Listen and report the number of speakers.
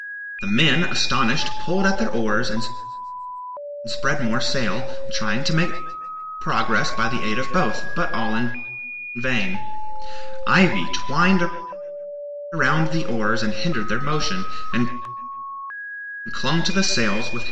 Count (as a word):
one